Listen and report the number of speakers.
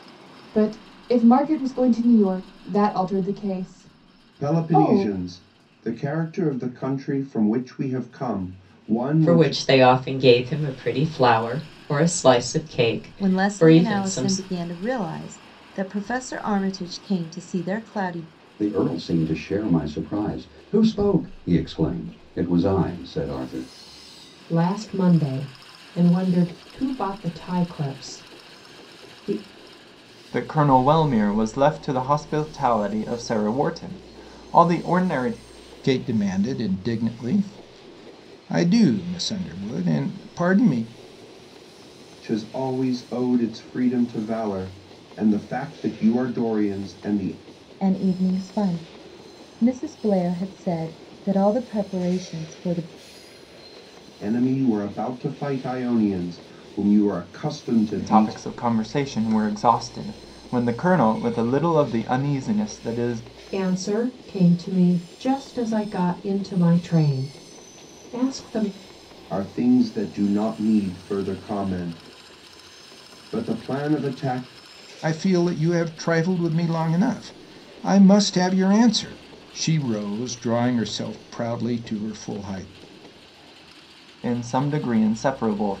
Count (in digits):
8